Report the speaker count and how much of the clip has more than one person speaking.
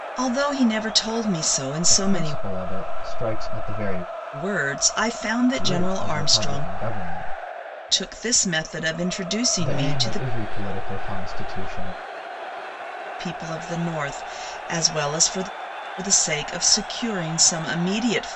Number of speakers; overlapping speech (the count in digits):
2, about 13%